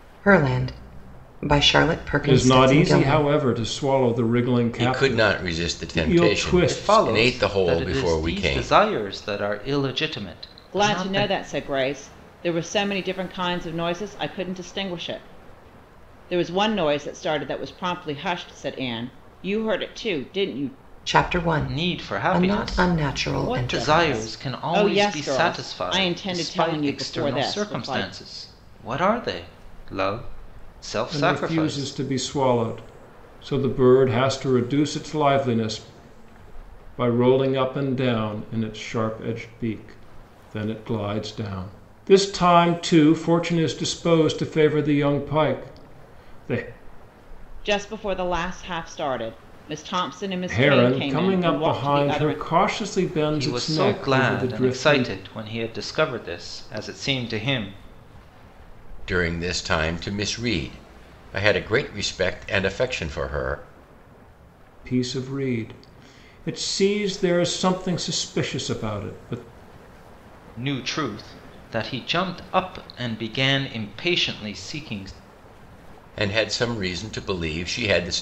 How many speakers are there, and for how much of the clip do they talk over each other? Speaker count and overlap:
five, about 22%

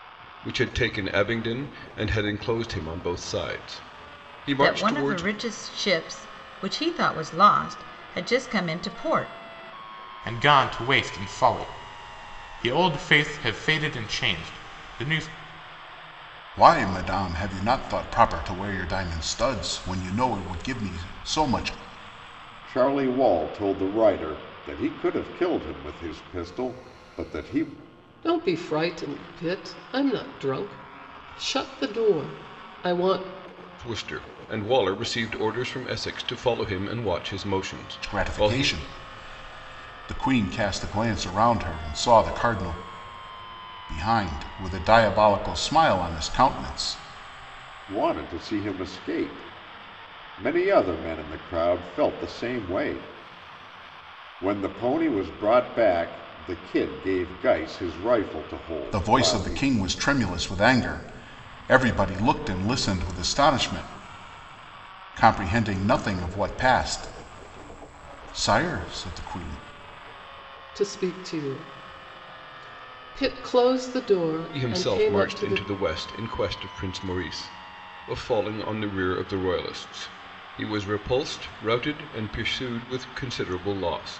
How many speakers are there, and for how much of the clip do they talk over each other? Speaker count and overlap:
six, about 4%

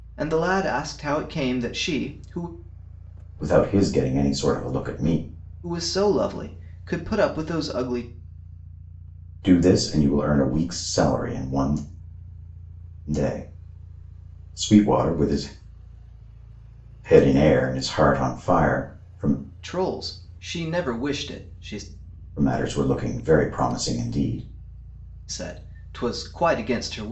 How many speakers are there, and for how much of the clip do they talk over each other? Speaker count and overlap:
two, no overlap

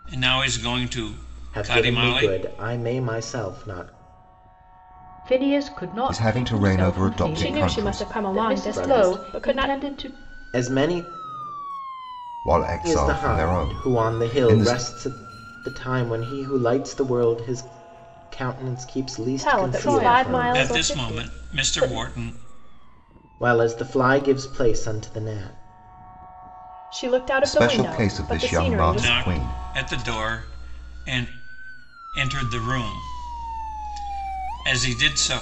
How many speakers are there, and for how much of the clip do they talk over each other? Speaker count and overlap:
five, about 32%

